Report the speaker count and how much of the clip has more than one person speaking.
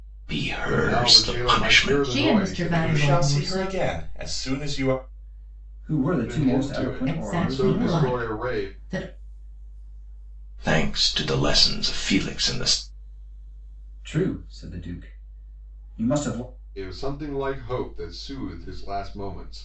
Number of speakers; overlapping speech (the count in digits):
5, about 28%